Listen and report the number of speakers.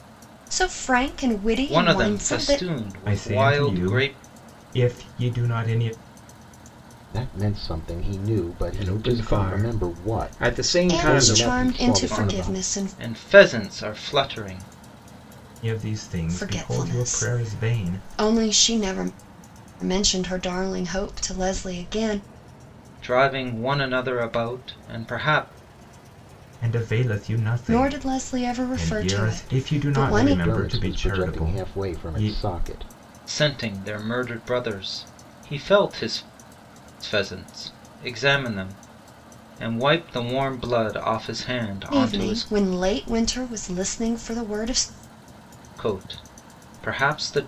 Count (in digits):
5